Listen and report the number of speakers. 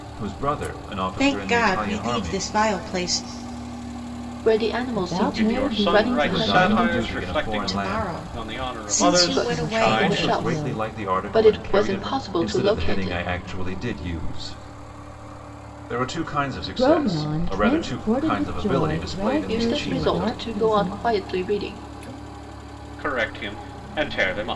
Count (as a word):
five